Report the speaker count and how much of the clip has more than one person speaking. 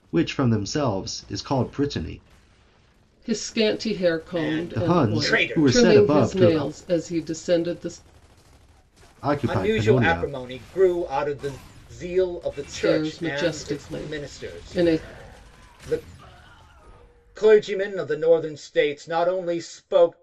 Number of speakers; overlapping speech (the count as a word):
three, about 27%